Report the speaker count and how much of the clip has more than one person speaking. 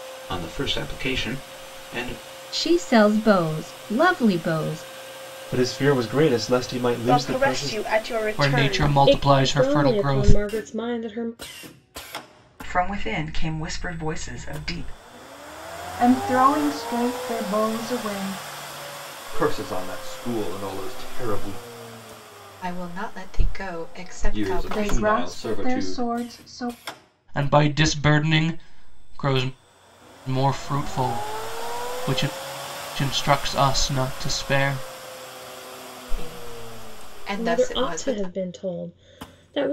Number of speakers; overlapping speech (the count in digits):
10, about 14%